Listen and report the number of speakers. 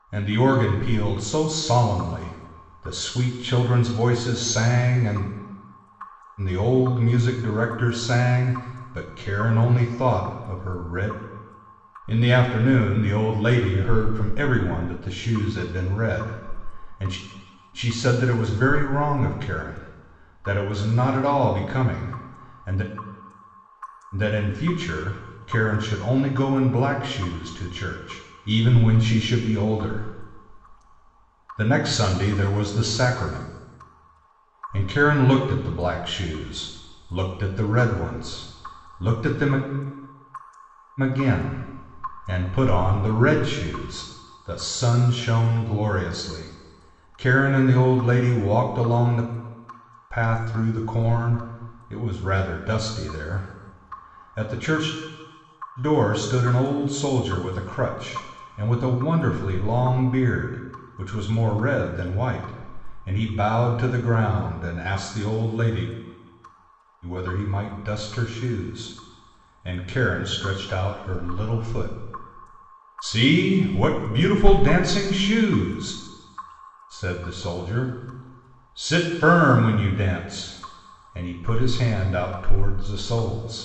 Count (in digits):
1